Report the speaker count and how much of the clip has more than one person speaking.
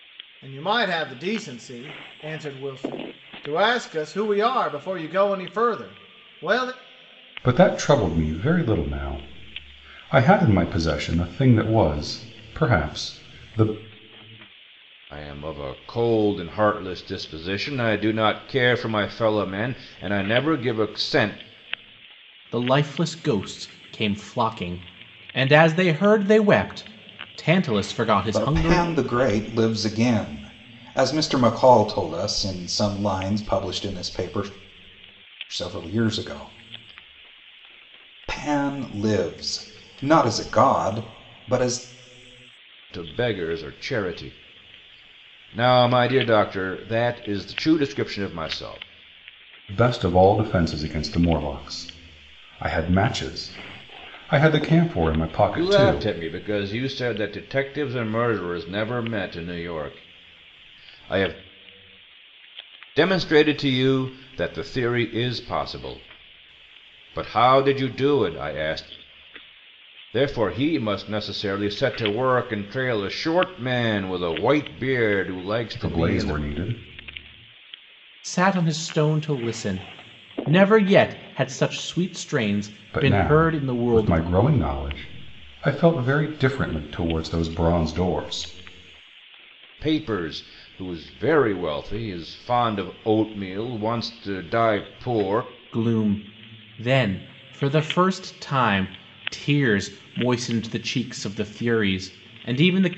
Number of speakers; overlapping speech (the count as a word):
five, about 3%